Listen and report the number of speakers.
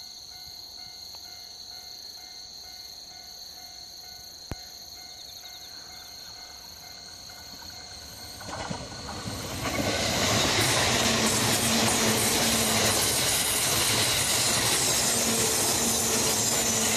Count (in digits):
0